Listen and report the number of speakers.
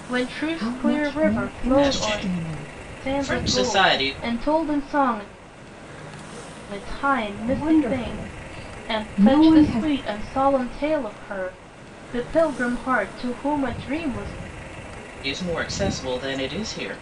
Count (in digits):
3